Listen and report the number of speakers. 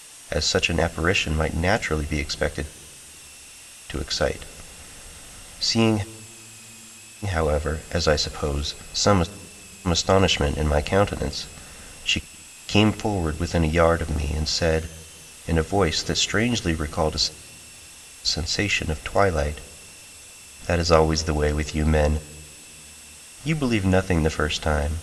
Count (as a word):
one